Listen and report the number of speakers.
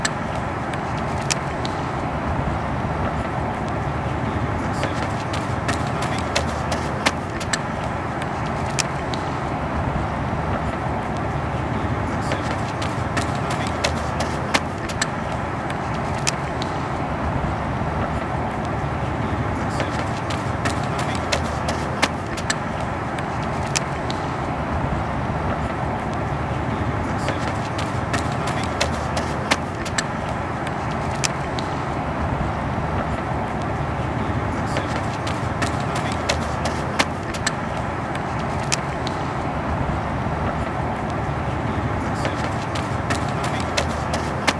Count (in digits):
0